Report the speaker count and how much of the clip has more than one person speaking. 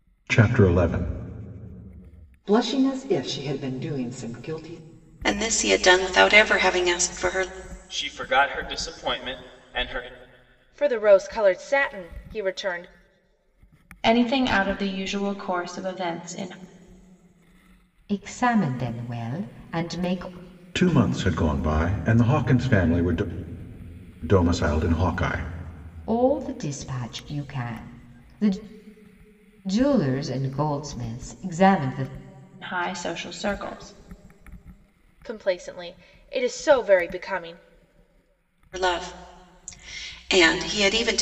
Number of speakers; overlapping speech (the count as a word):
seven, no overlap